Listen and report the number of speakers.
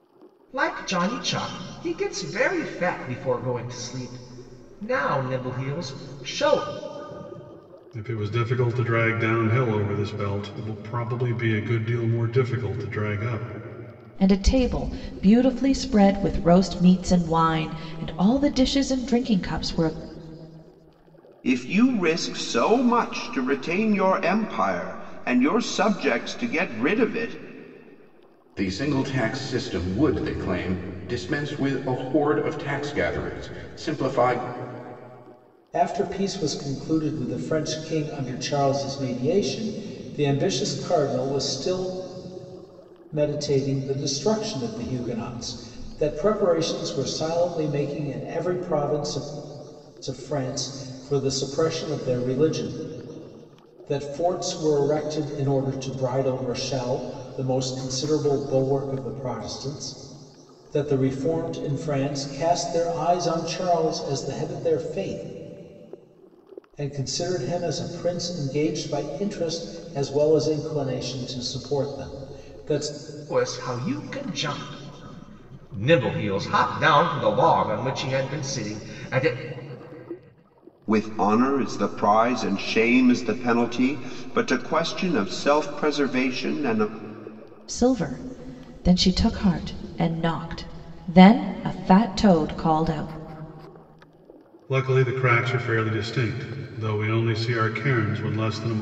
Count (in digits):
6